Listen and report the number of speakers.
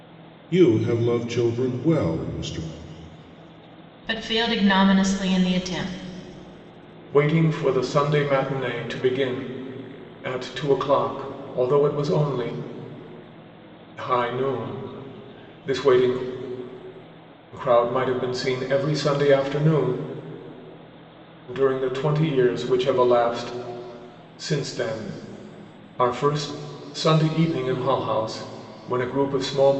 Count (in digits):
3